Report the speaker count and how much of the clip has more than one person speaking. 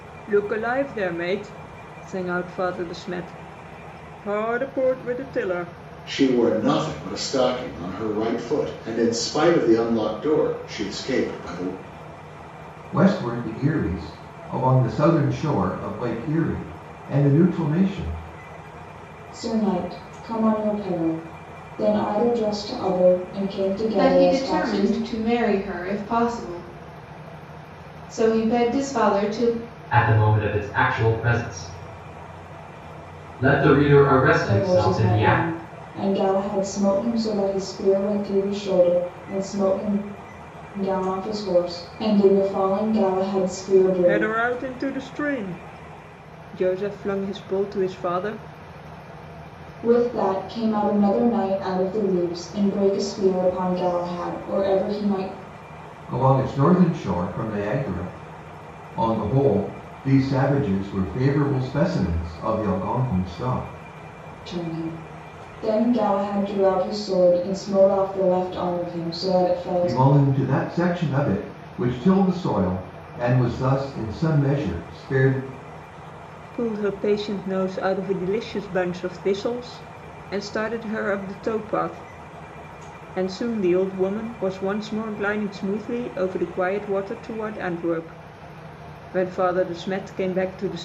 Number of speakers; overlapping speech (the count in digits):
6, about 3%